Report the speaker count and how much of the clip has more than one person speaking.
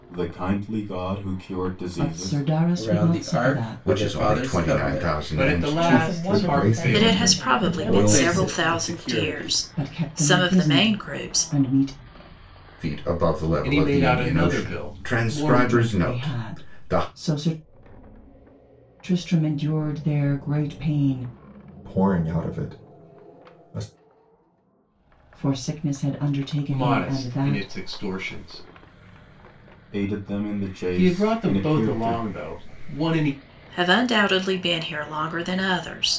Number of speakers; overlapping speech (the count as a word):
eight, about 41%